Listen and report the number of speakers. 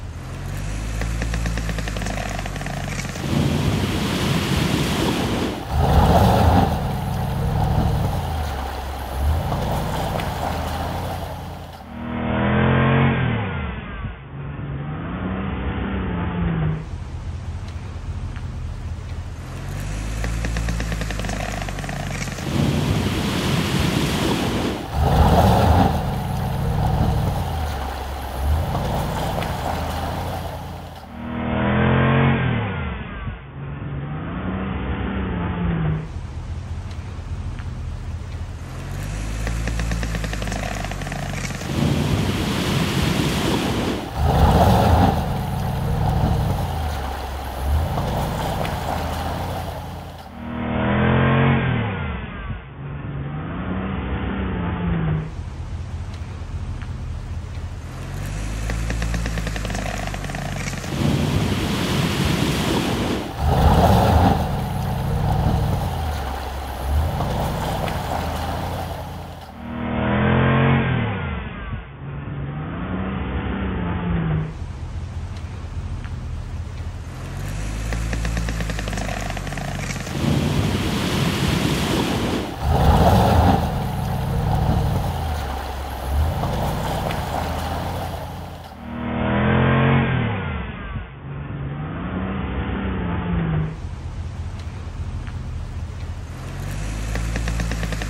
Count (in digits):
0